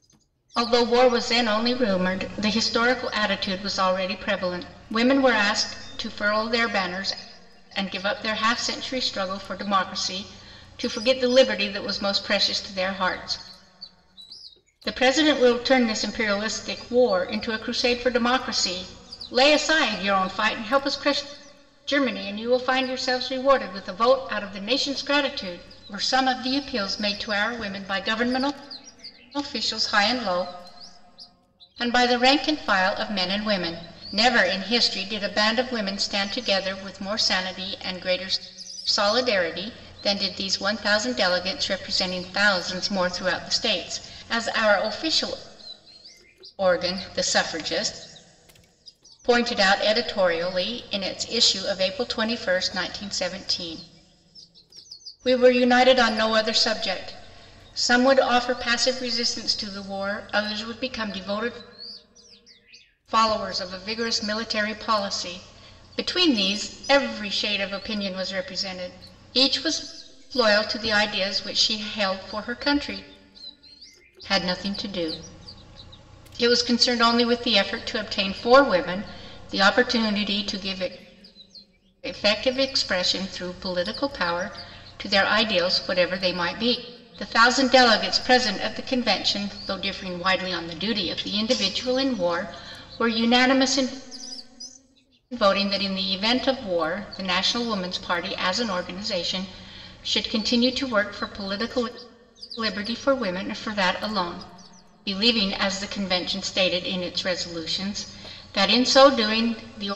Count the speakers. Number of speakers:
1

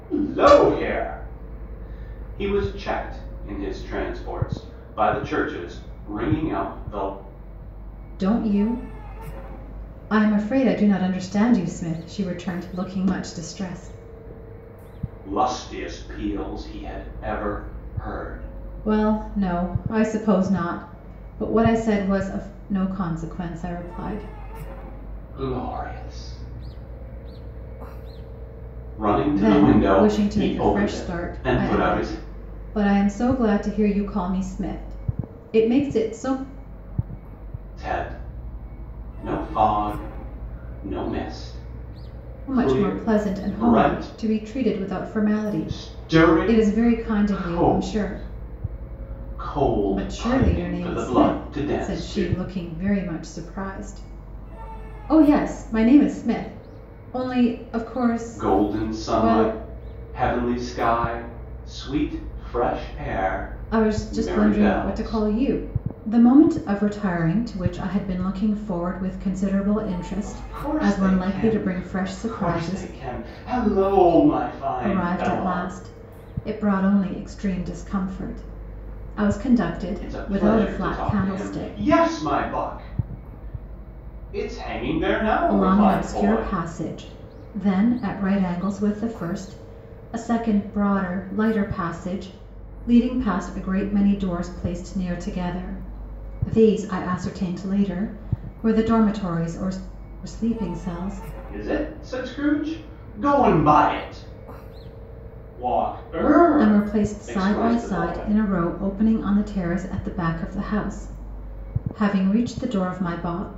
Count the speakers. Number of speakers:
2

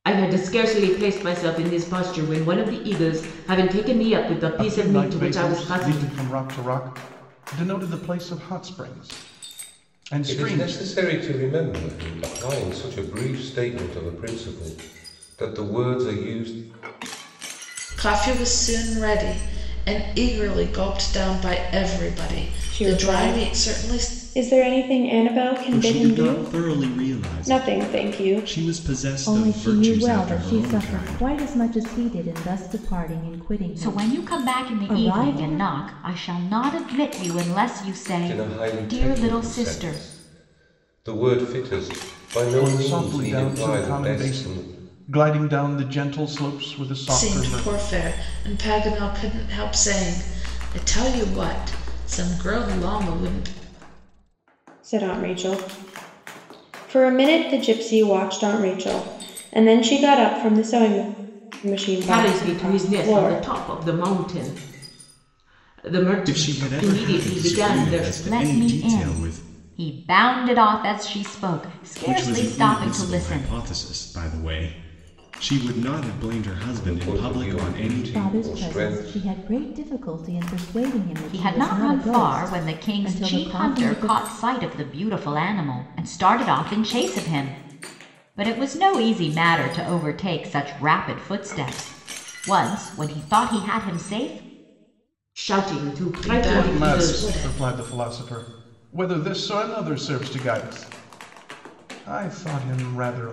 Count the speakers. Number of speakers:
8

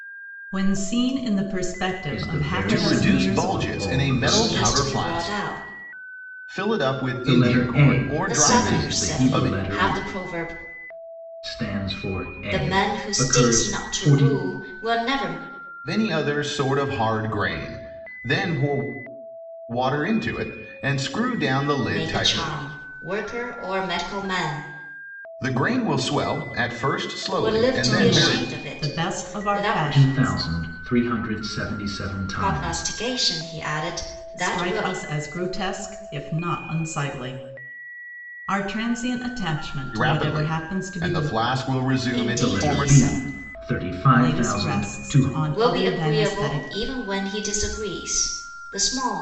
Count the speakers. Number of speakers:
4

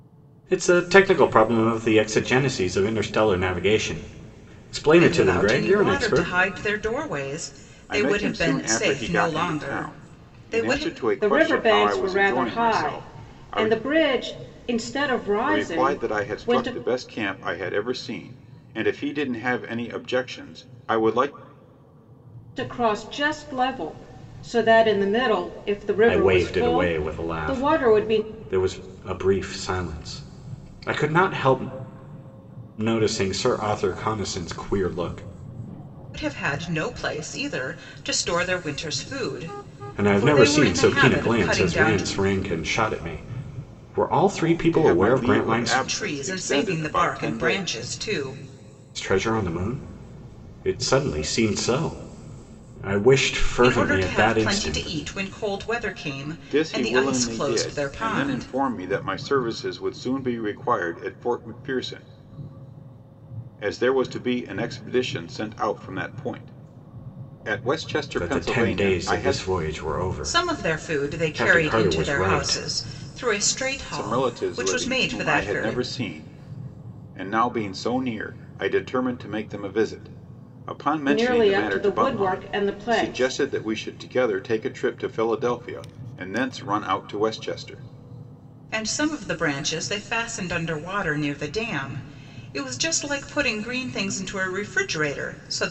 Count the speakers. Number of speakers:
4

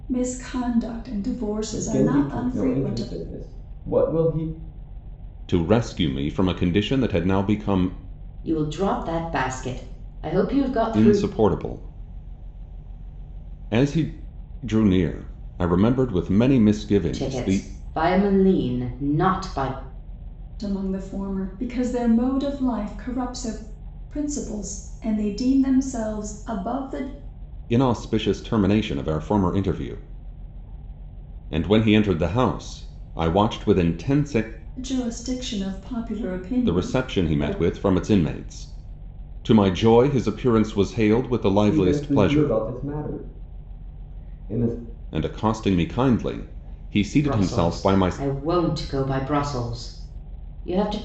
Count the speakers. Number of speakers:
4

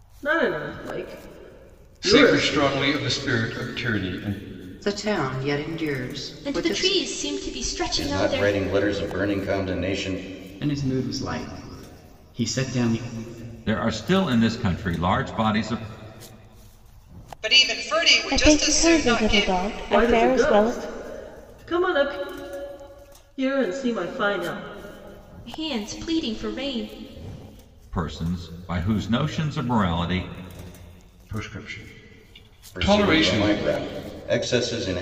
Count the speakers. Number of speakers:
9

